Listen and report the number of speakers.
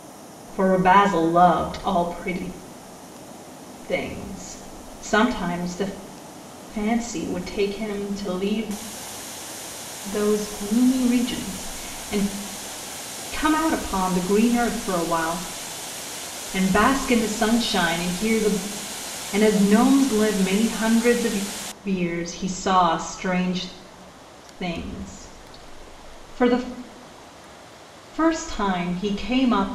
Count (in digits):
1